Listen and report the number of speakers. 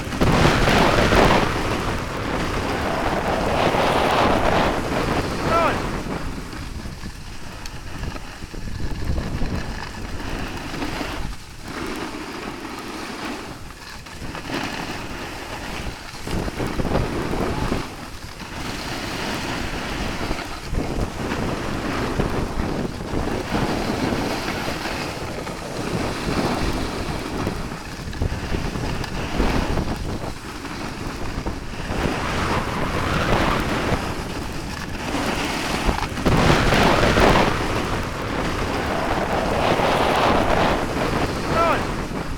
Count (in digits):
0